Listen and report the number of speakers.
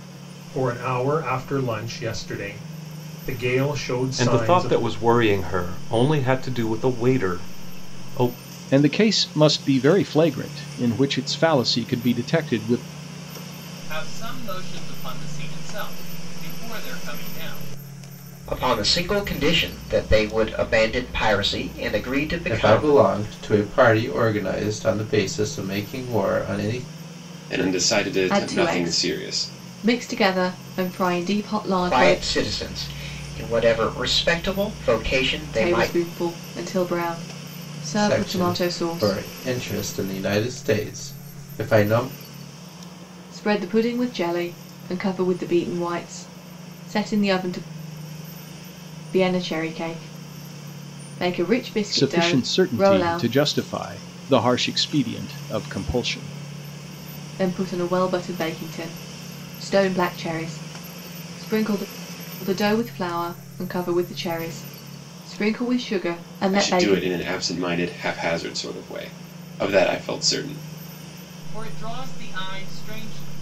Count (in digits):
8